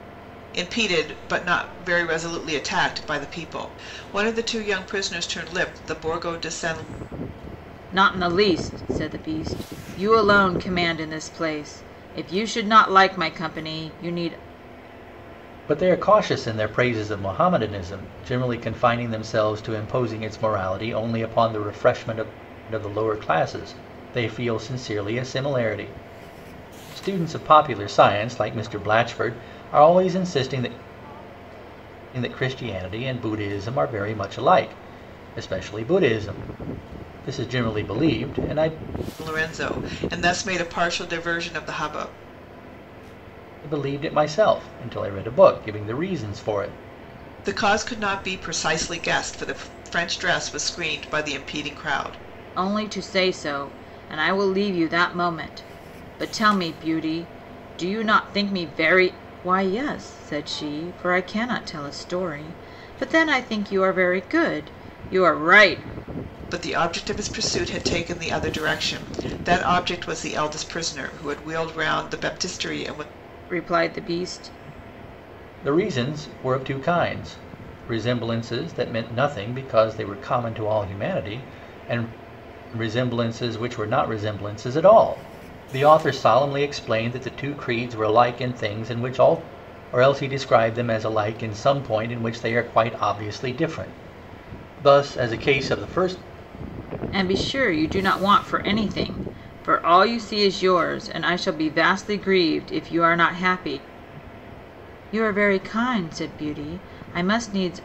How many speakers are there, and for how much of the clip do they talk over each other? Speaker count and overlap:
3, no overlap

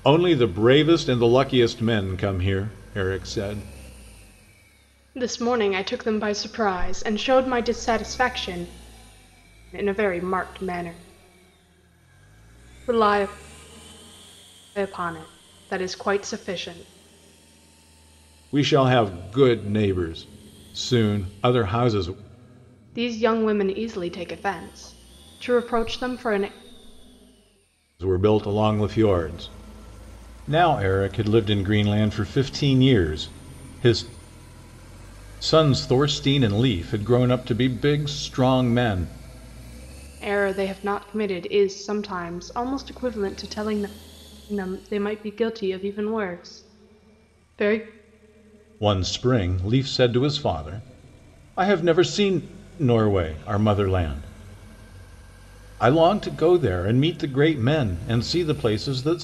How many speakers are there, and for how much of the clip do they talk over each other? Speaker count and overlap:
2, no overlap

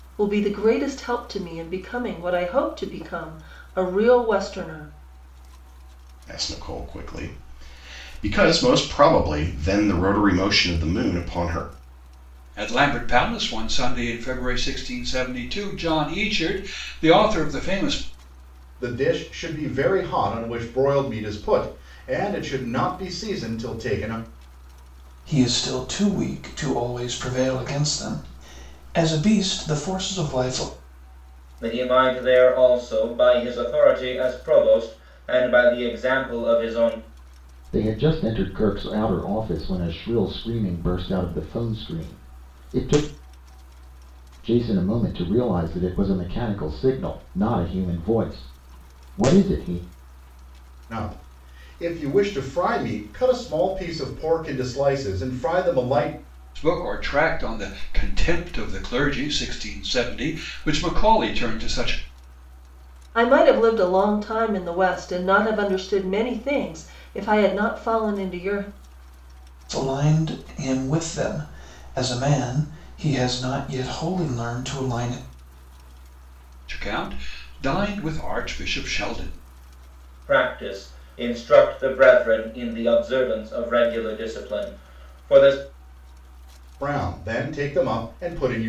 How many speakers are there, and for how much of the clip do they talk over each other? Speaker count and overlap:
7, no overlap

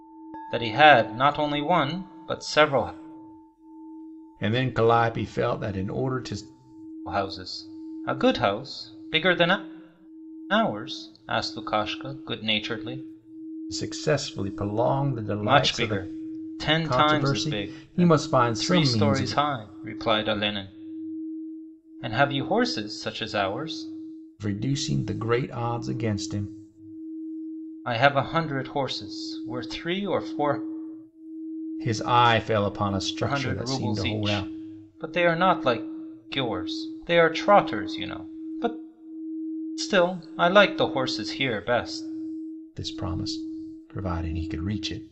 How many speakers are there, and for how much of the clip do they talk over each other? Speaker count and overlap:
2, about 10%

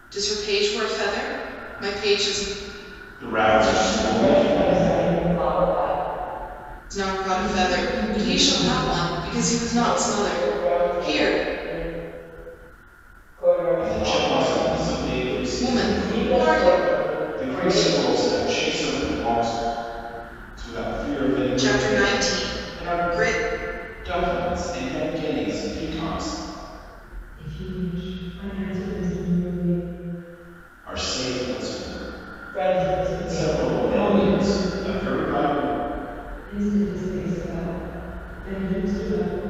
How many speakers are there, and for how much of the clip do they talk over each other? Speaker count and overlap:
4, about 34%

